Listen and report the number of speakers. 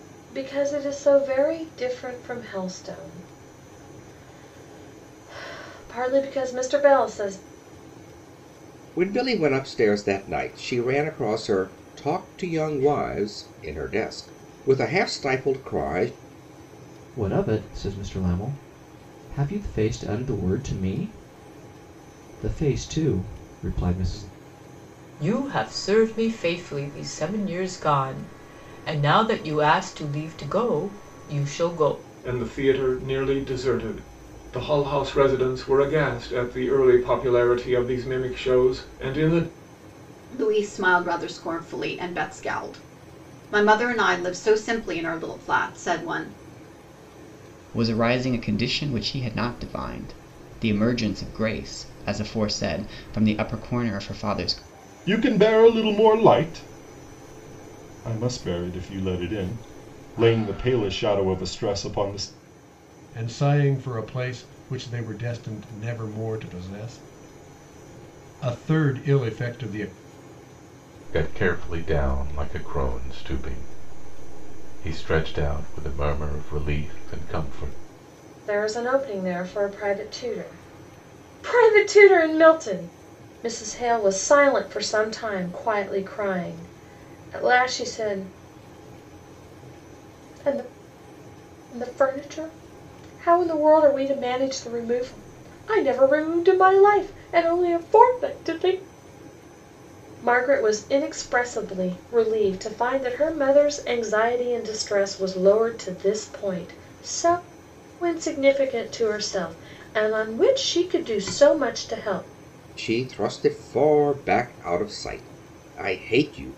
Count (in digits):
10